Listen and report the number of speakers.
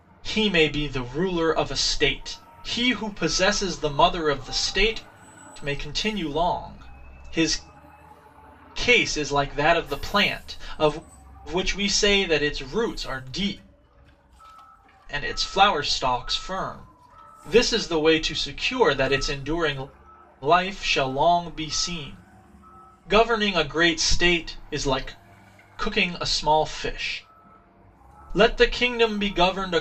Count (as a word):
one